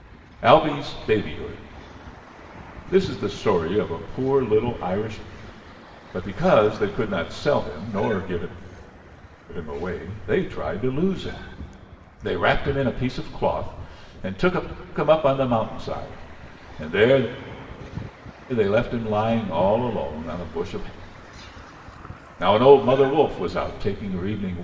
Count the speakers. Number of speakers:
1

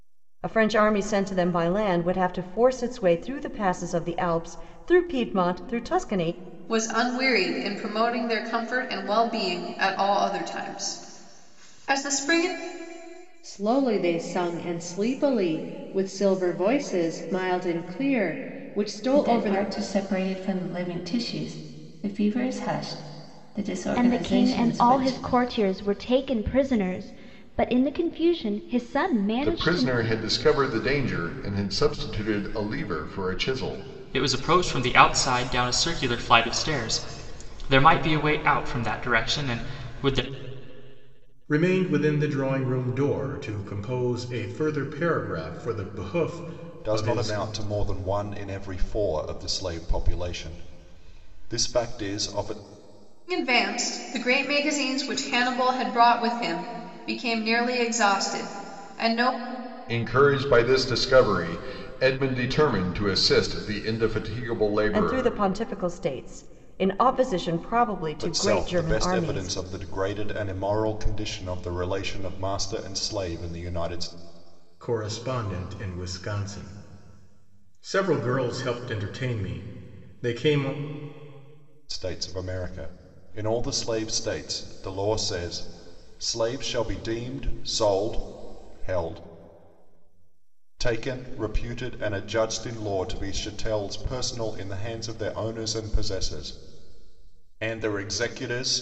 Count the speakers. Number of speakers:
9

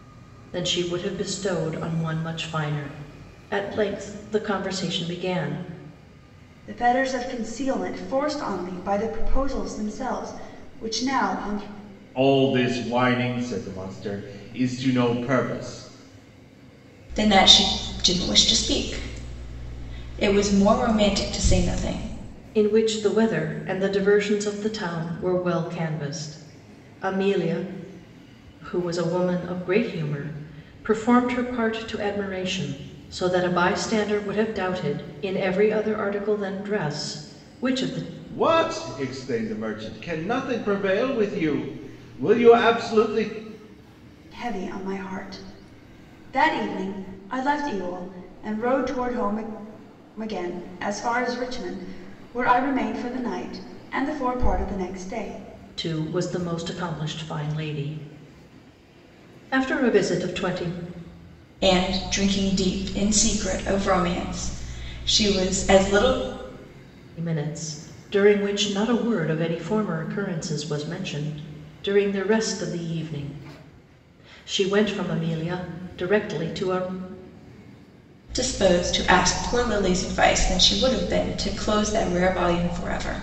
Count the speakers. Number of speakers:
4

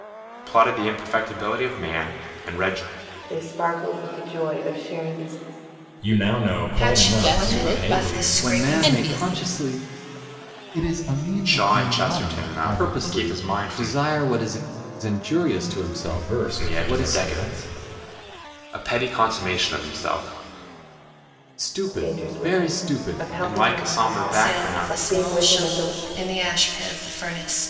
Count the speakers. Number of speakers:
7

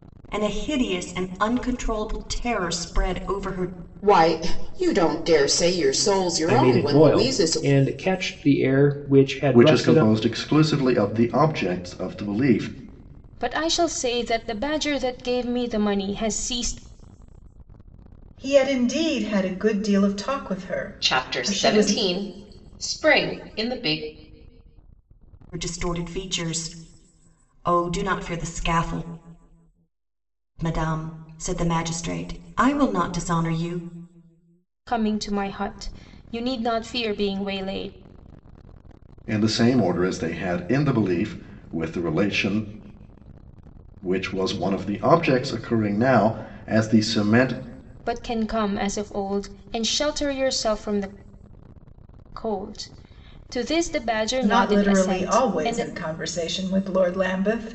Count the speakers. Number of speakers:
7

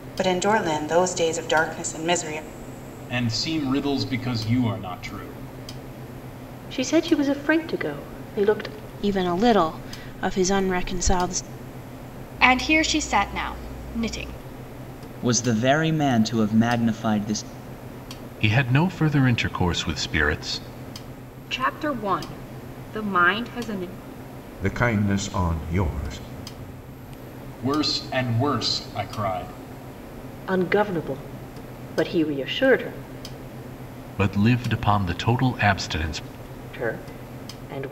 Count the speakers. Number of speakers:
9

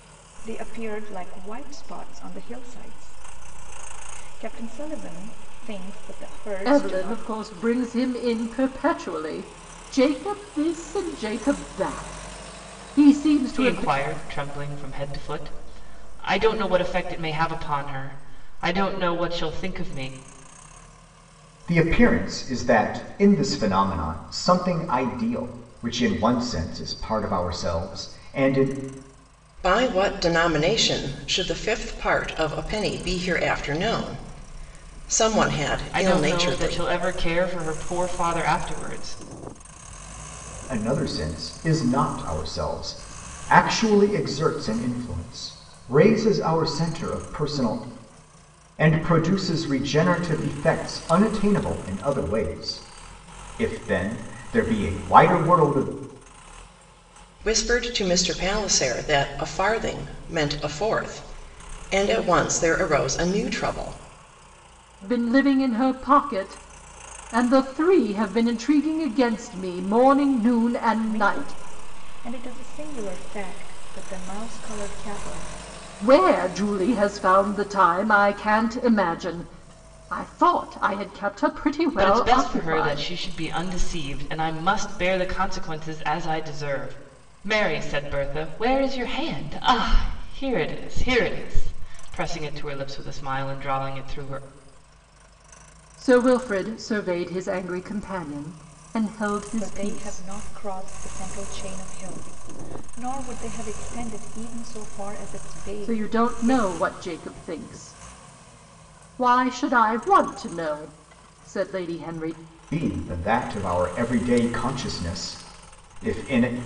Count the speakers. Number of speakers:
5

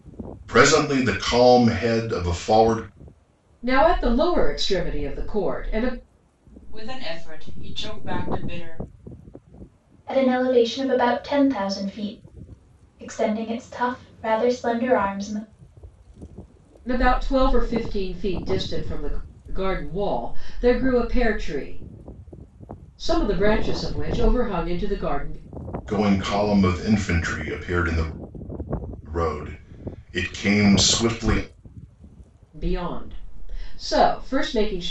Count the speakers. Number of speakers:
4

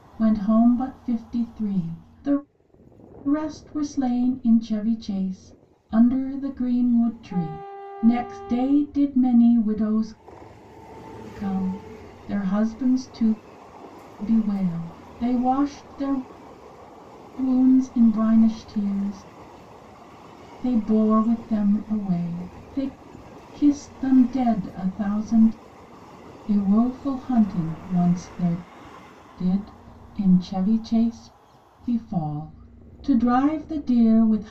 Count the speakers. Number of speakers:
1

